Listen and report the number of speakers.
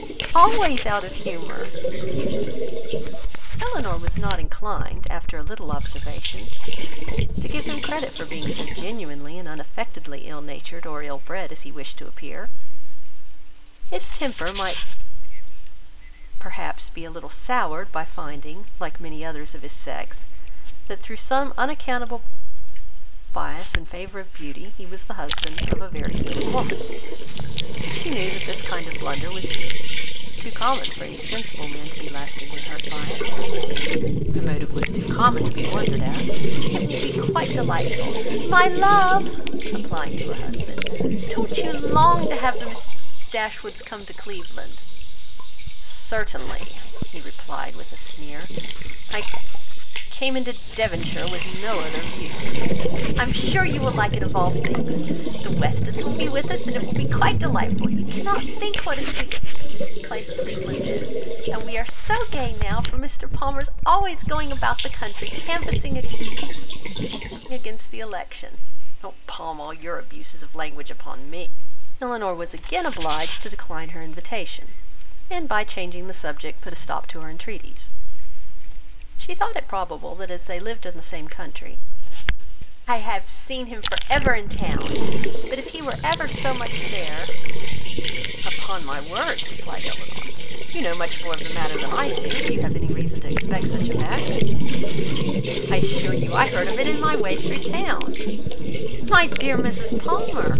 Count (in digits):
1